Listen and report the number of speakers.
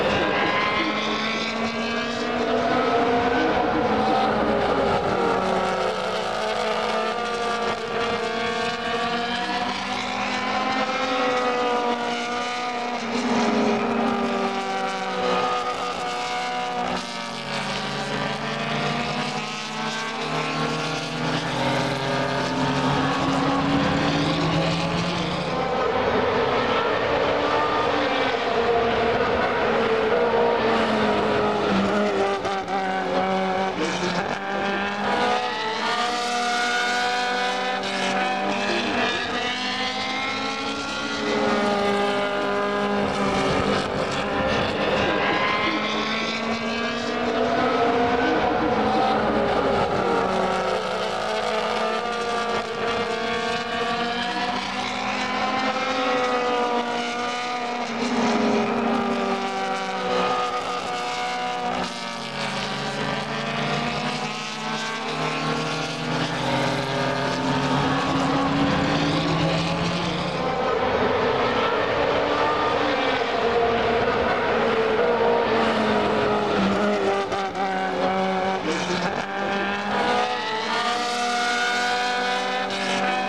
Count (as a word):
zero